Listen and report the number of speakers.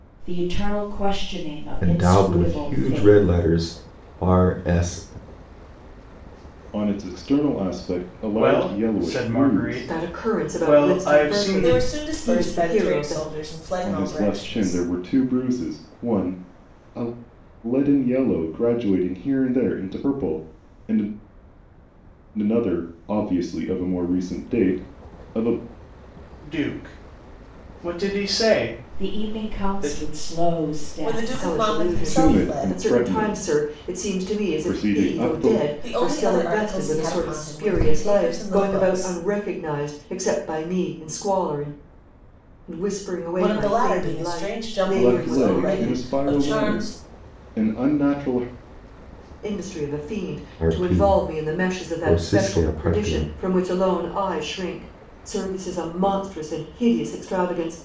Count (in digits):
6